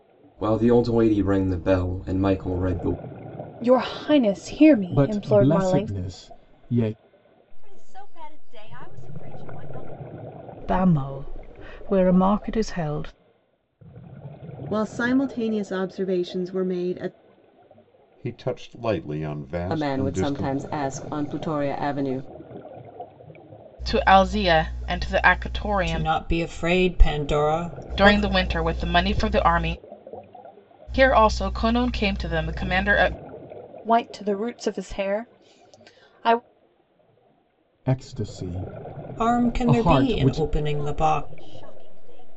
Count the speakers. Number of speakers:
10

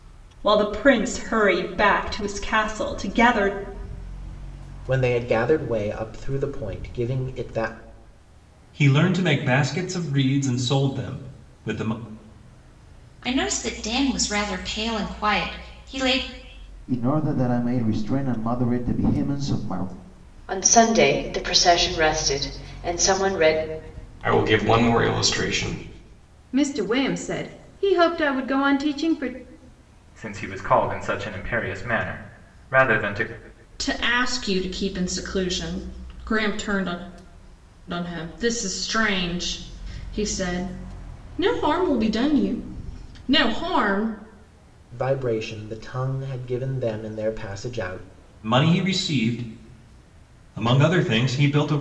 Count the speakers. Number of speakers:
10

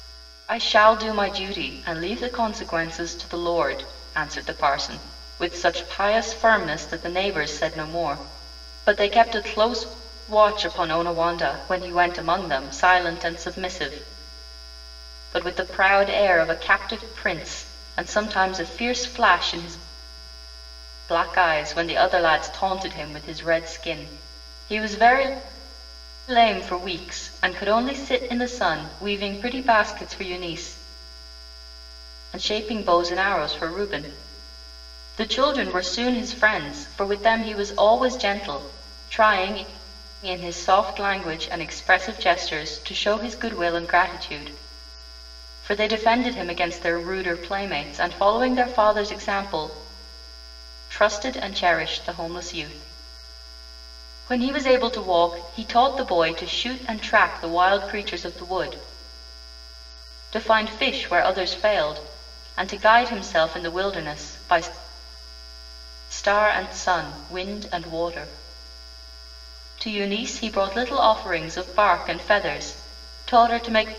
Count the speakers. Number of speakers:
1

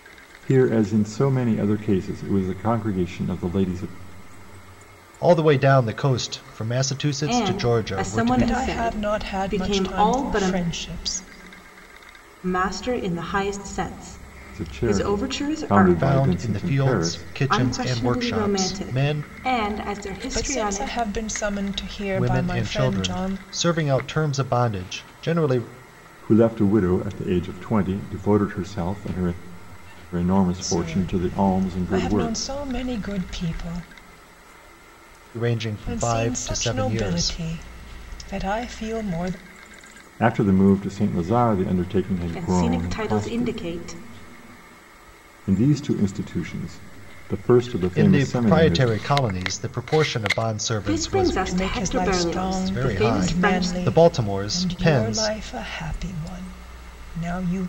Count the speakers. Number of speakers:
4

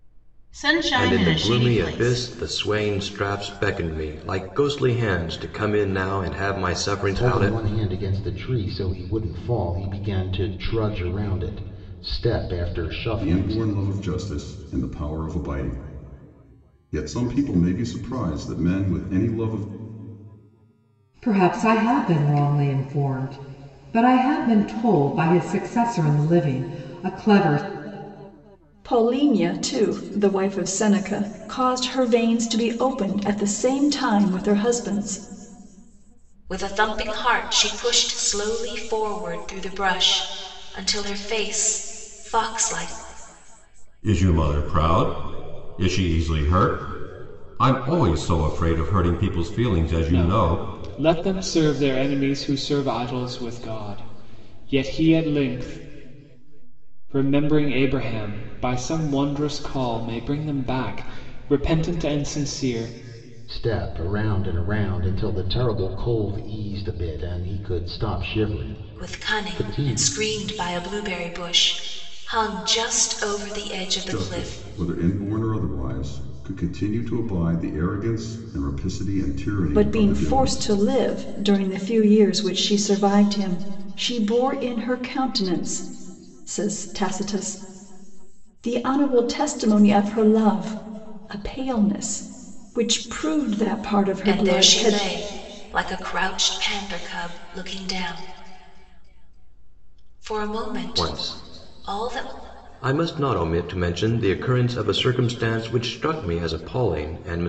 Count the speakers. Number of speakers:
9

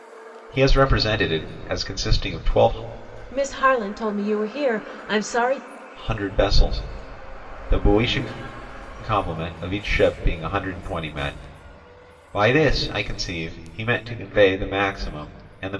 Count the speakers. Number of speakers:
2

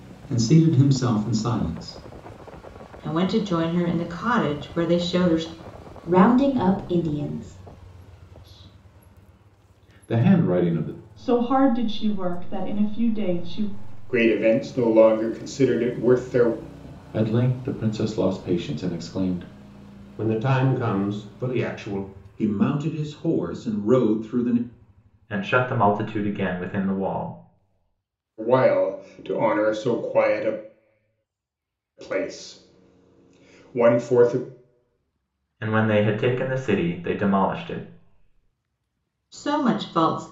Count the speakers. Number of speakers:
10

